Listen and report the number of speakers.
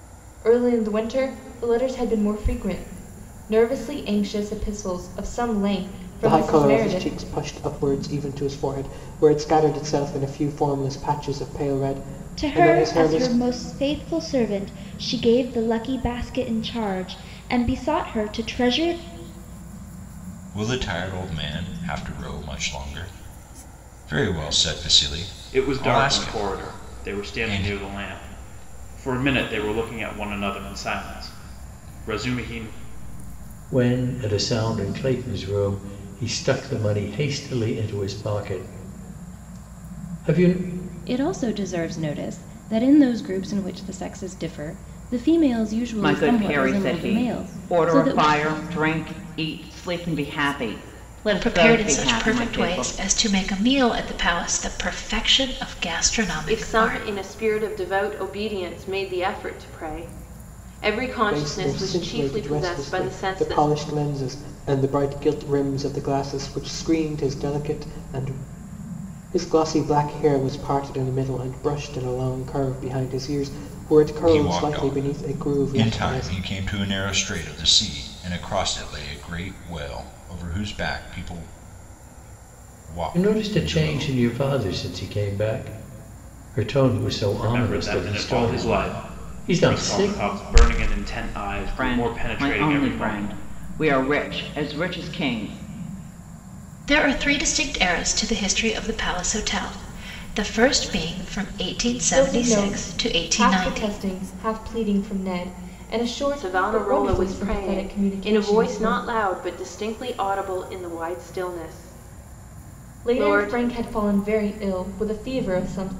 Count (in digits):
10